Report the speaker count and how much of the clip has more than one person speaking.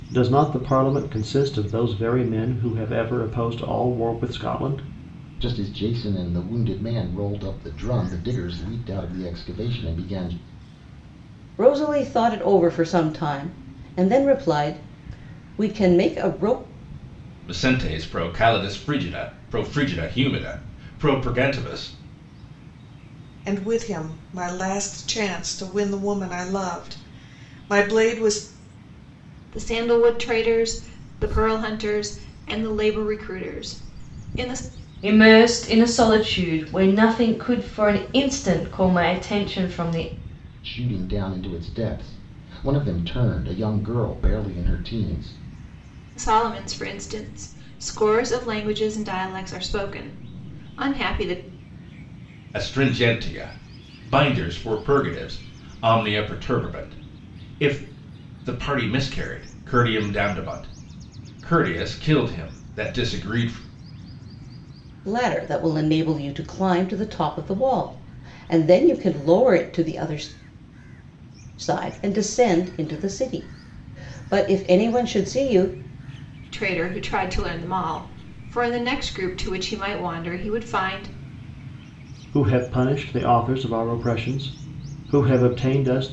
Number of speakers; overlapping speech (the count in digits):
7, no overlap